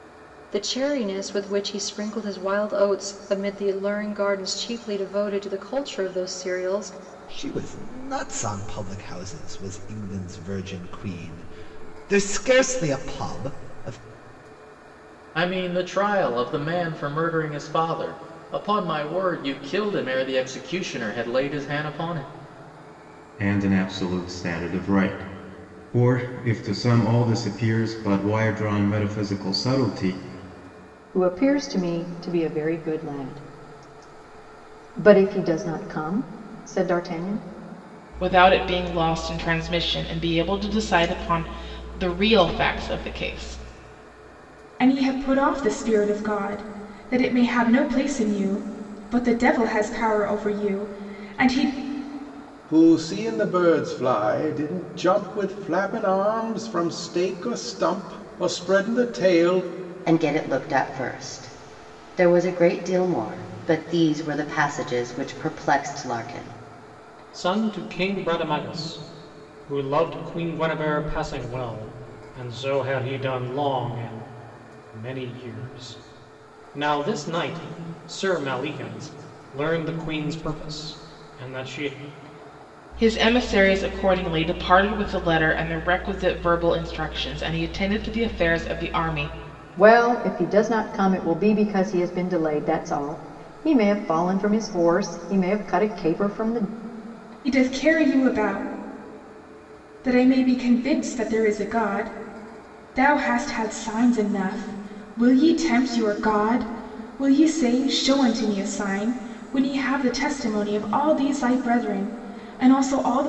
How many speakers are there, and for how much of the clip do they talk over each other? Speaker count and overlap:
ten, no overlap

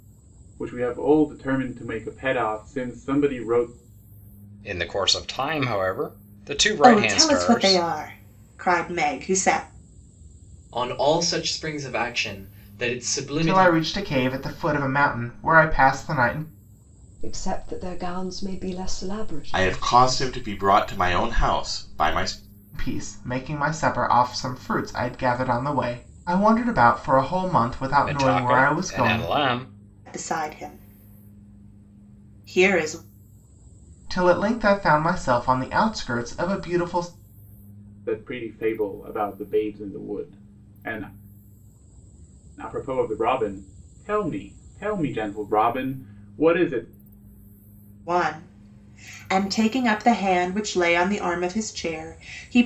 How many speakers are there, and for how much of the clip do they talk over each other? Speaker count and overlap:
seven, about 7%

